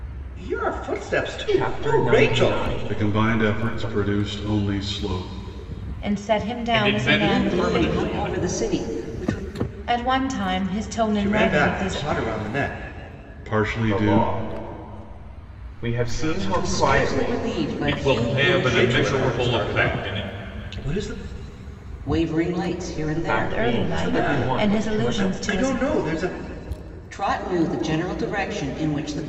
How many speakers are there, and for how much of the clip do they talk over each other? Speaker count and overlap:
6, about 45%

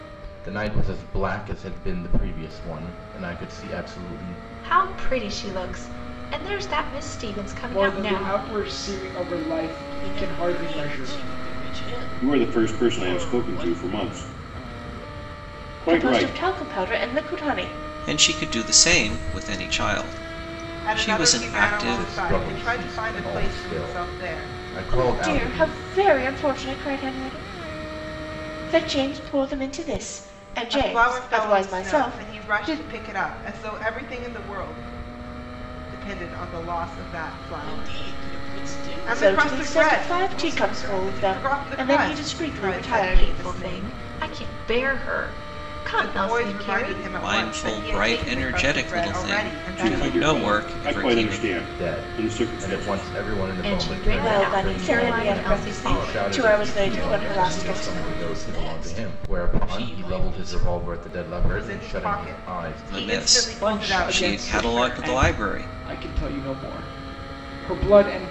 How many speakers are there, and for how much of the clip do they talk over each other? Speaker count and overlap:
8, about 52%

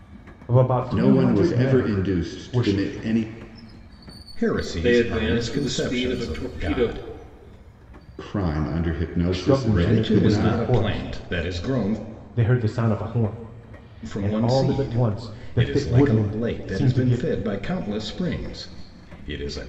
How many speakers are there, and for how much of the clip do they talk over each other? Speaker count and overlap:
4, about 45%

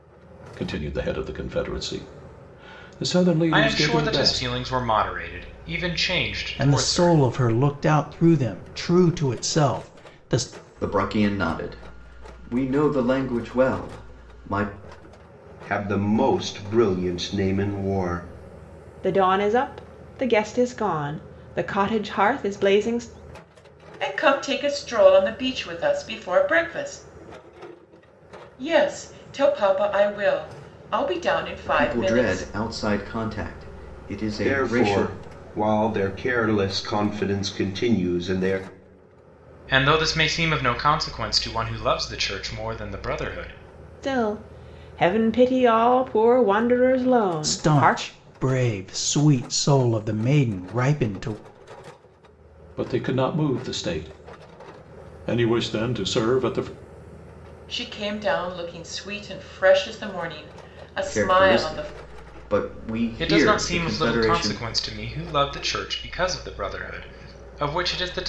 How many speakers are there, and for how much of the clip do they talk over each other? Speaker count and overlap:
7, about 9%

